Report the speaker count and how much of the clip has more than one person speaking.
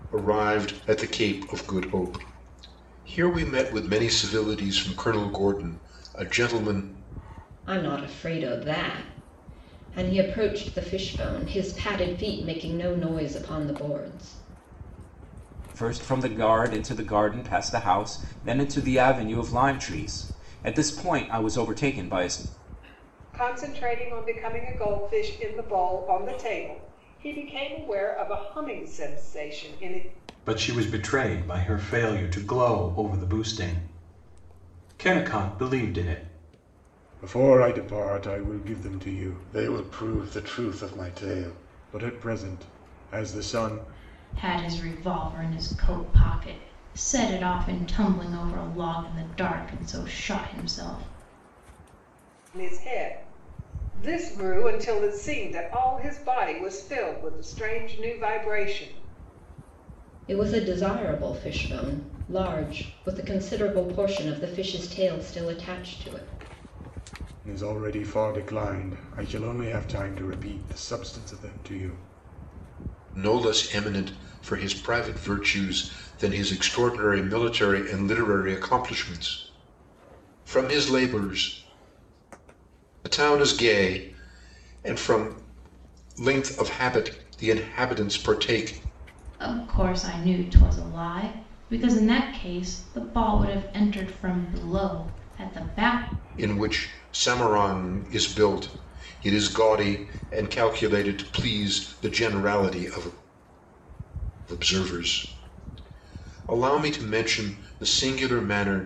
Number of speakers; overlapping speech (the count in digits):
7, no overlap